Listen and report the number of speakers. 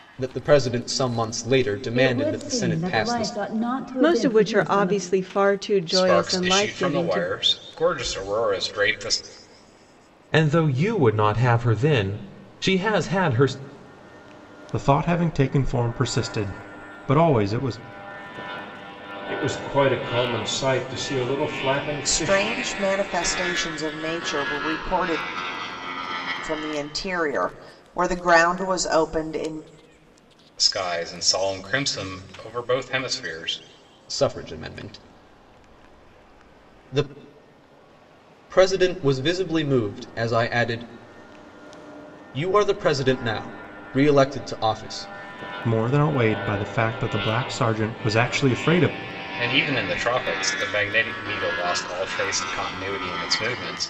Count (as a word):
eight